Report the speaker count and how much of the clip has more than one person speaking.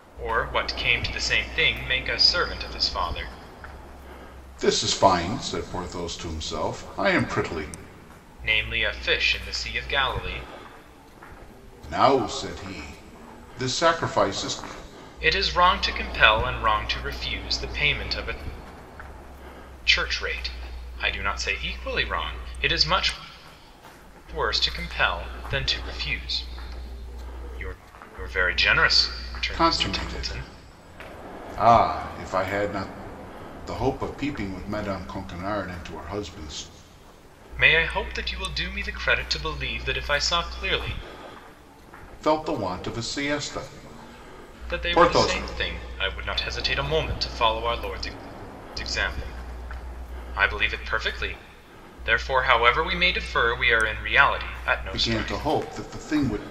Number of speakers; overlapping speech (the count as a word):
two, about 4%